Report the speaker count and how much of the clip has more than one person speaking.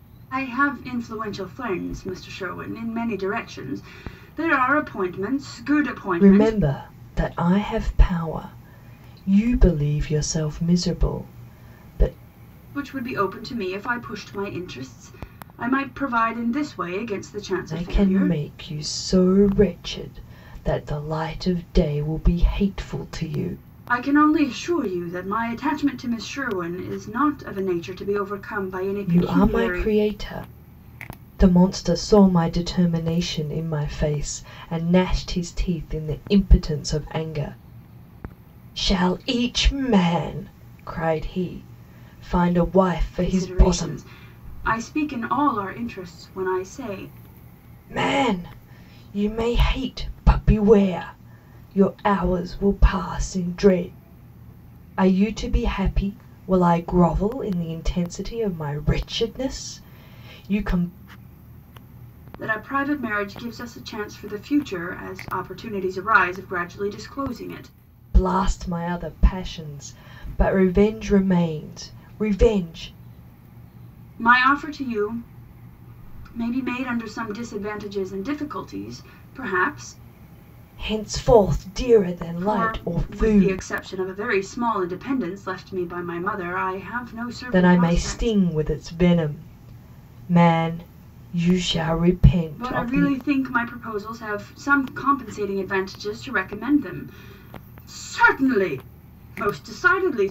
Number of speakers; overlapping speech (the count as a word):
two, about 6%